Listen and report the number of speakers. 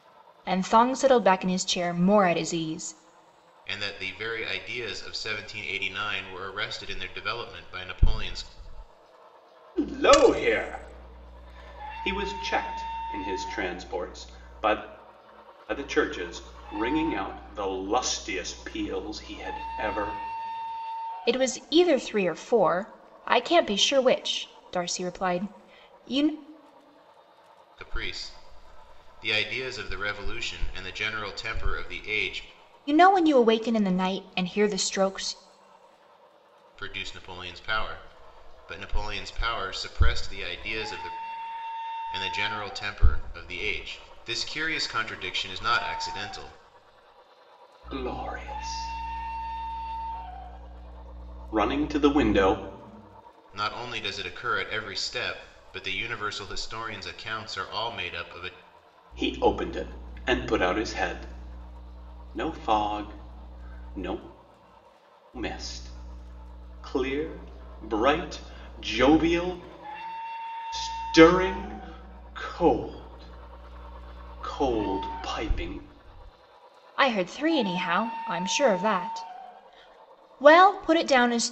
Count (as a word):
three